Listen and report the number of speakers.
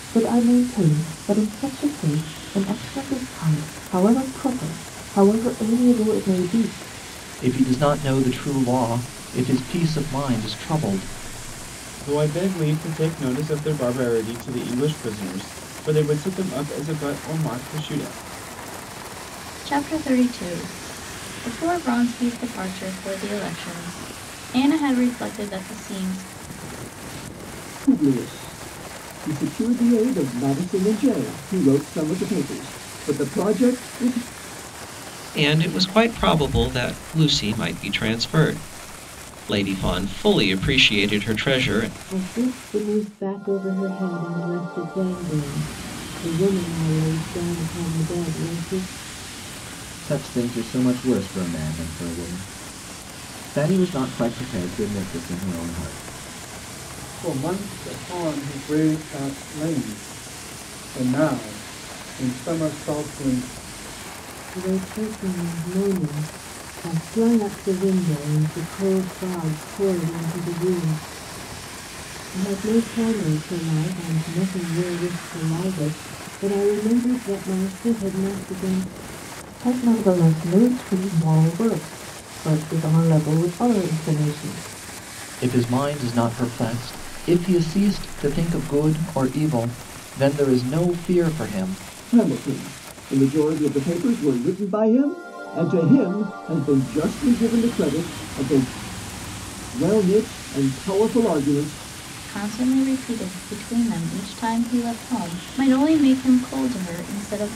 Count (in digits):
9